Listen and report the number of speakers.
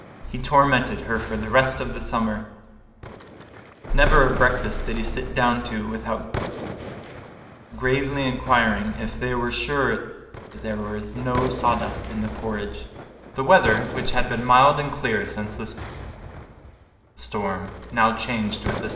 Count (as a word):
one